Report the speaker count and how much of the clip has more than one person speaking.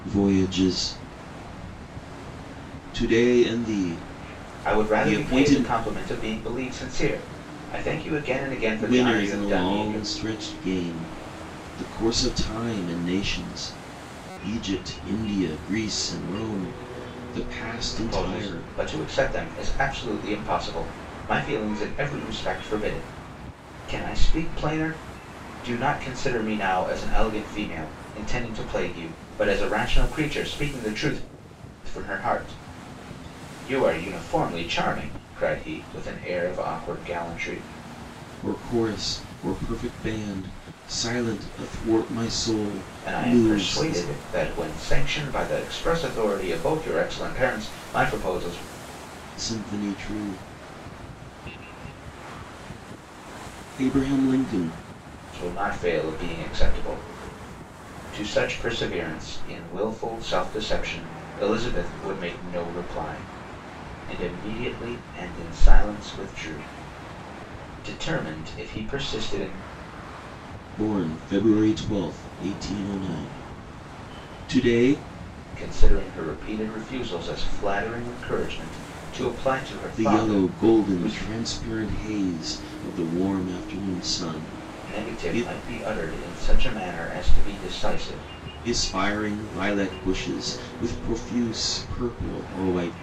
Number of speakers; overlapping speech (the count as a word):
two, about 7%